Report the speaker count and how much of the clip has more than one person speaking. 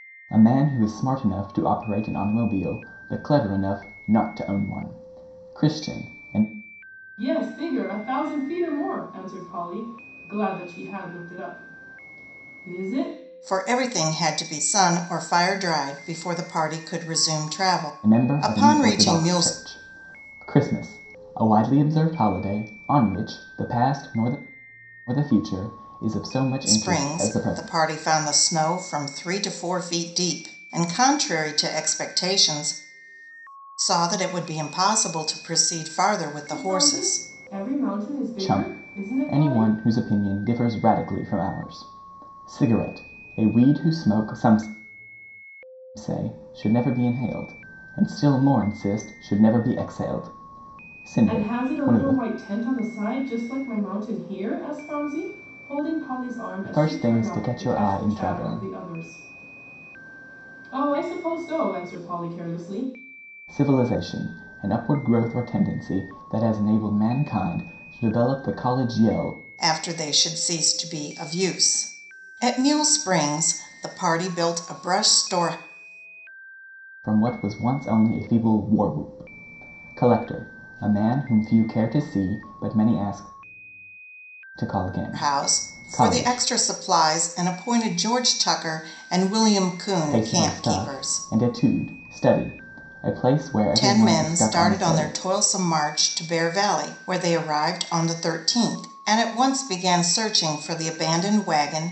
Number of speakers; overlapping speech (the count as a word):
three, about 12%